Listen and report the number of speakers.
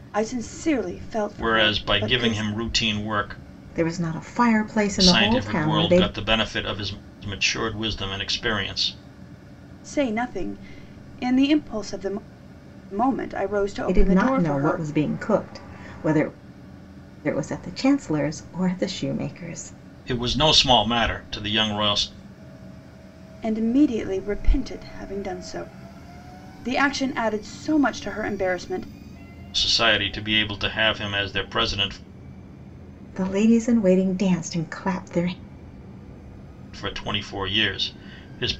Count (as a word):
three